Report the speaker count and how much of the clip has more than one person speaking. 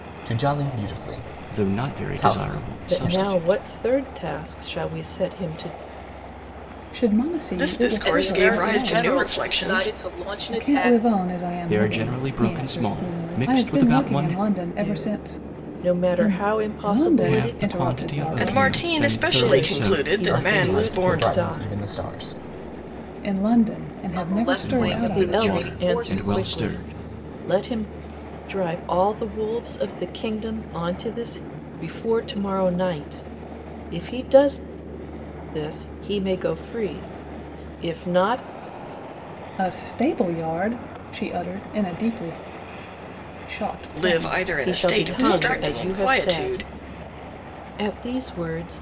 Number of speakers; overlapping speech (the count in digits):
6, about 42%